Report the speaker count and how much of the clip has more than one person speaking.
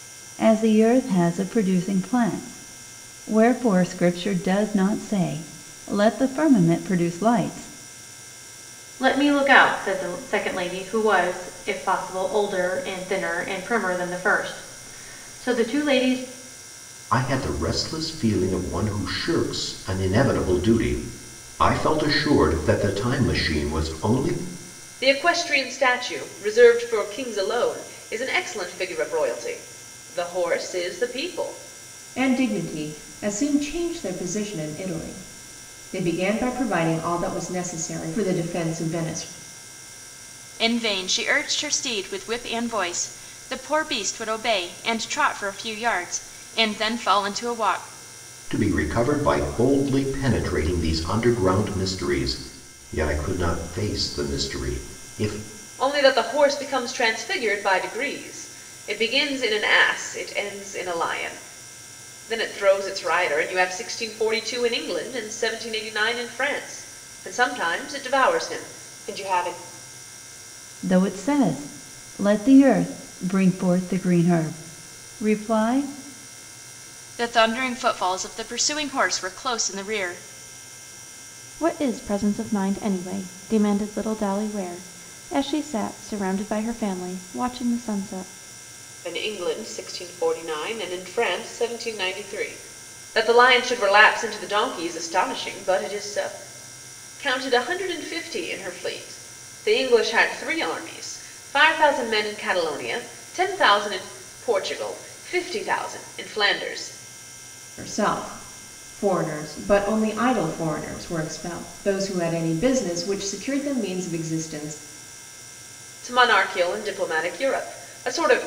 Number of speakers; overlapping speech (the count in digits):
6, no overlap